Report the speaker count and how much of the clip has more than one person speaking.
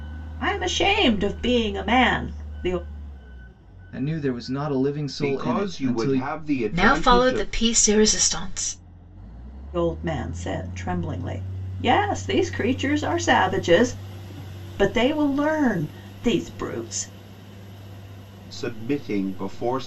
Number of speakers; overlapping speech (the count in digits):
4, about 10%